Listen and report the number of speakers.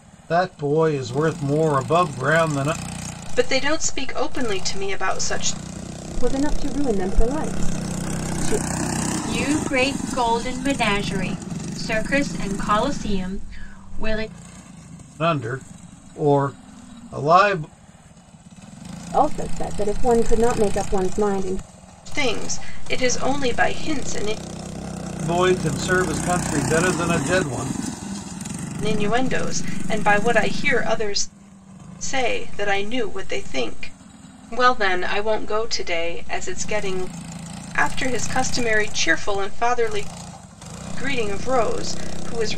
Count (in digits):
4